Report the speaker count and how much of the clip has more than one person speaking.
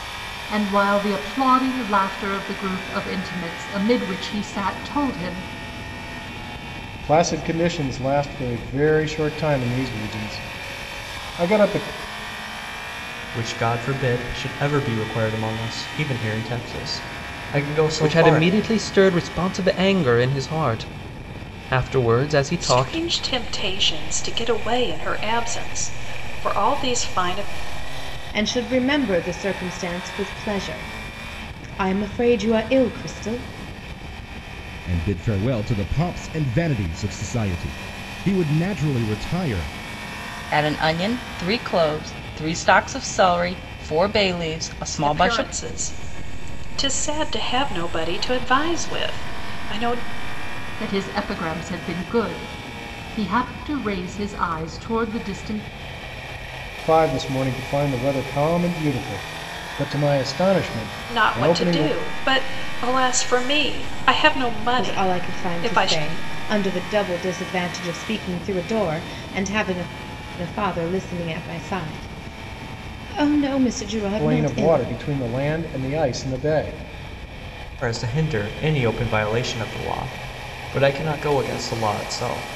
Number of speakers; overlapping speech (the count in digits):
8, about 5%